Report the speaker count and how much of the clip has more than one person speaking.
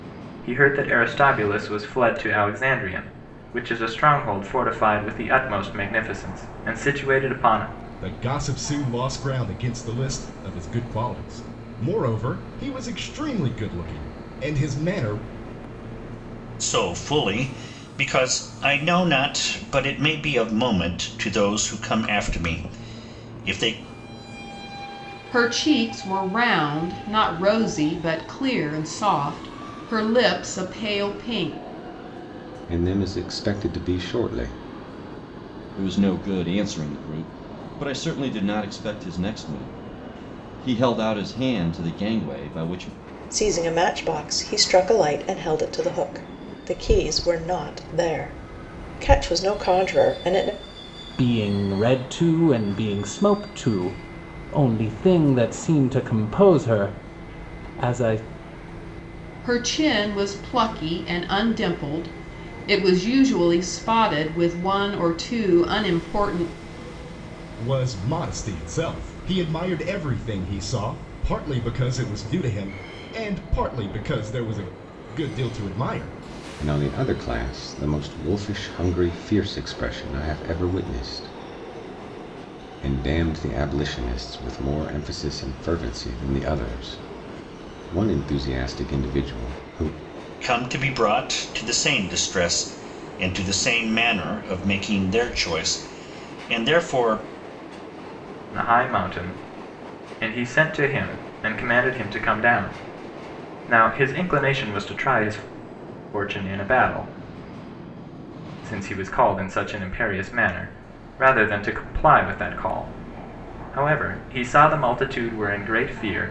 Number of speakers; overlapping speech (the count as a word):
eight, no overlap